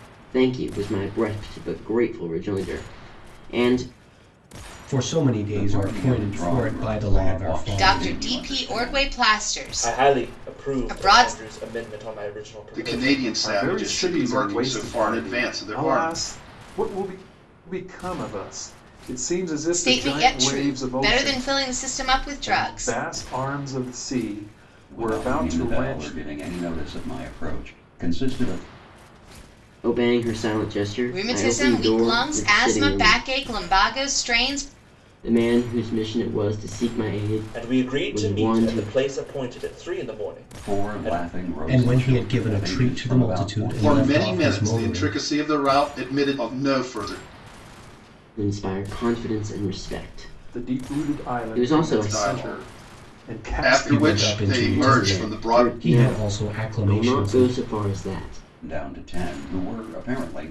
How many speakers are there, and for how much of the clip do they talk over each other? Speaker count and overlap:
seven, about 44%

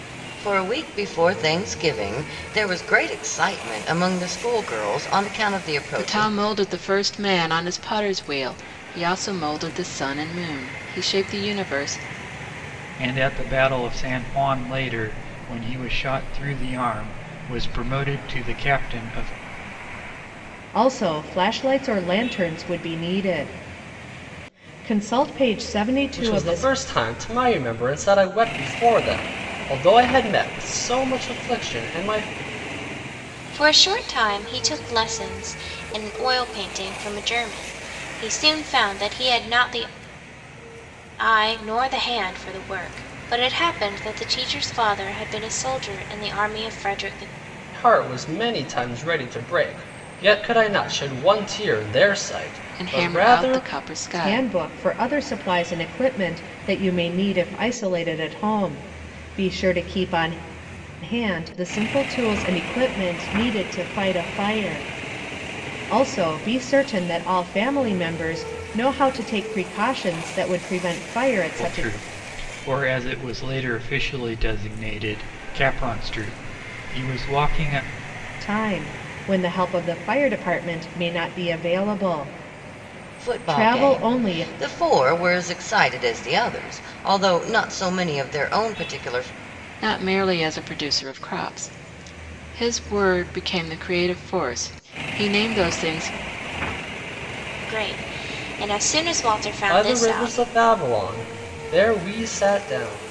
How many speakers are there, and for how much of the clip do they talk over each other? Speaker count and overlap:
six, about 5%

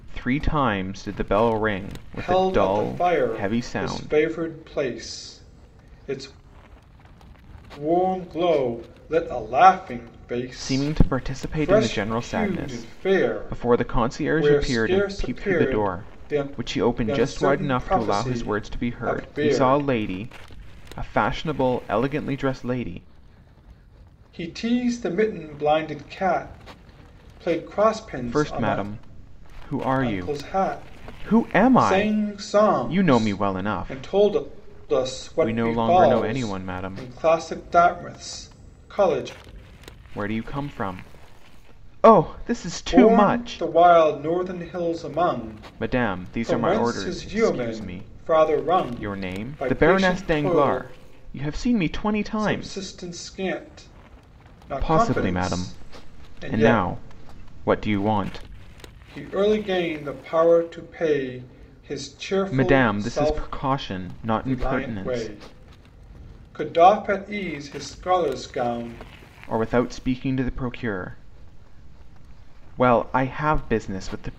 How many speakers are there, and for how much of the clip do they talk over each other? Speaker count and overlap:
two, about 37%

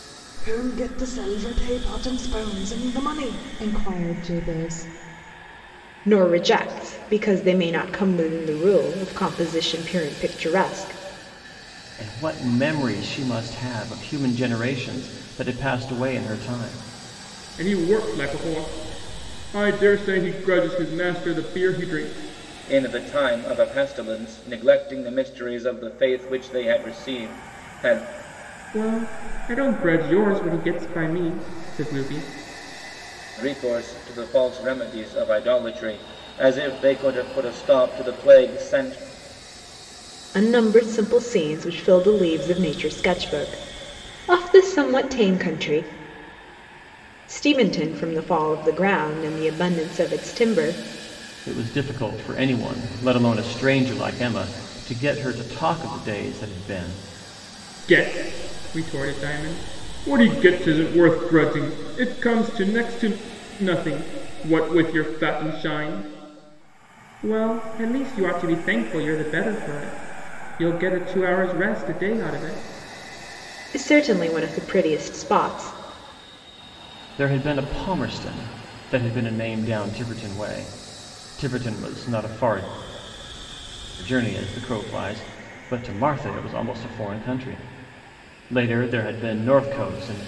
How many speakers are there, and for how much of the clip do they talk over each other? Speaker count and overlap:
five, no overlap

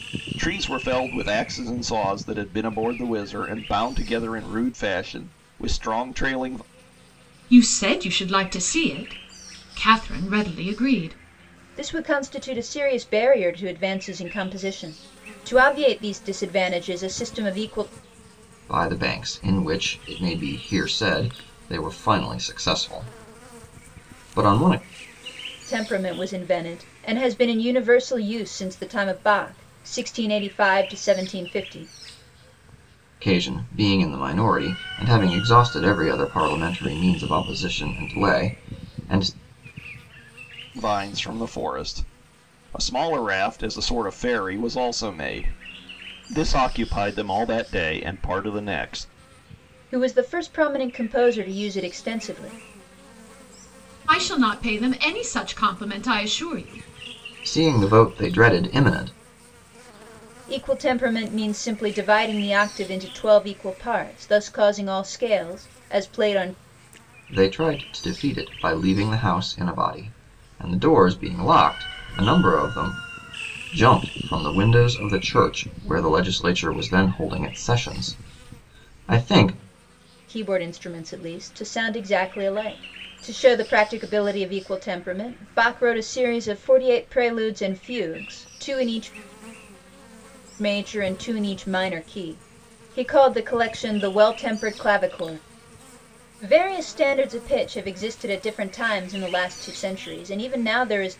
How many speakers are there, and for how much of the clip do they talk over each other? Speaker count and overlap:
four, no overlap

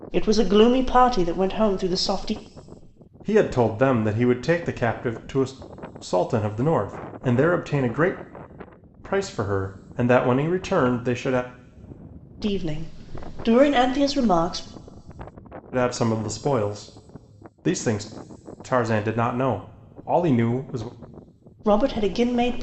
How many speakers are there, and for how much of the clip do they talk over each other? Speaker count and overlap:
two, no overlap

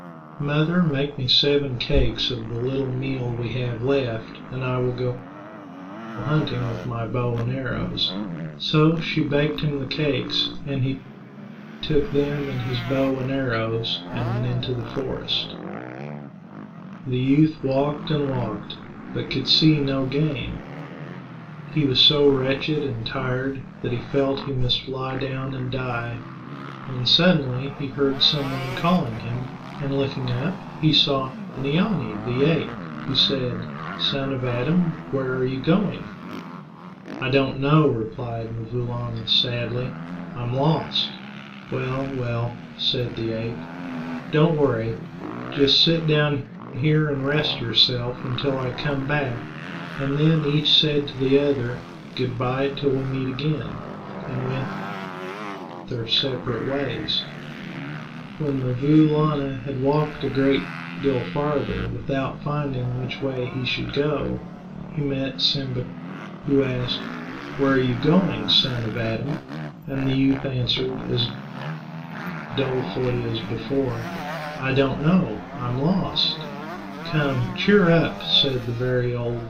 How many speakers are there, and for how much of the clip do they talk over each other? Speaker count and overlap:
one, no overlap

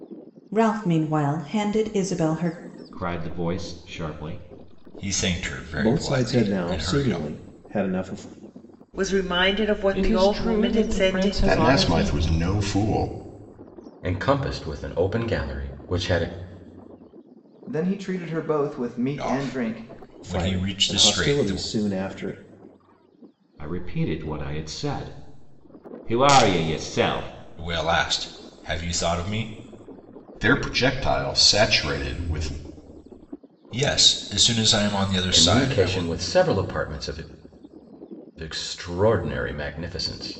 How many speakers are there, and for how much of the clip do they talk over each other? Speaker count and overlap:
nine, about 16%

